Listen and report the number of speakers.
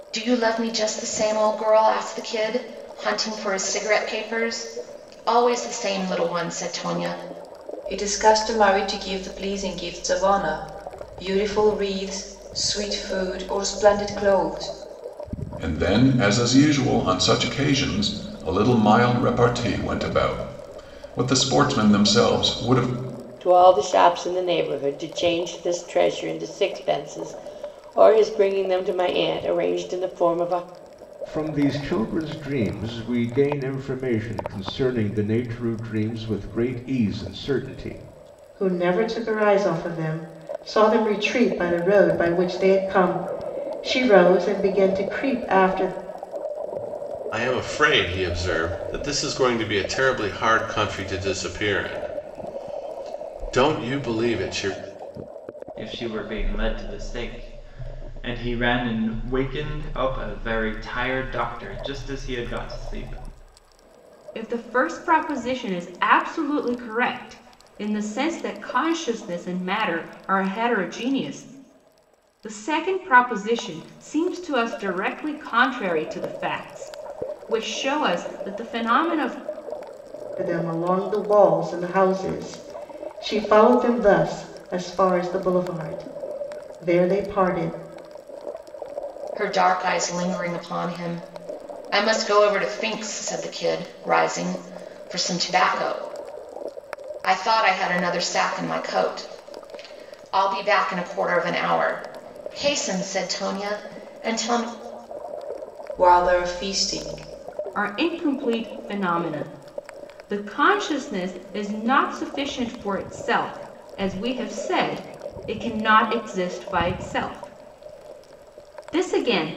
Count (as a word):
nine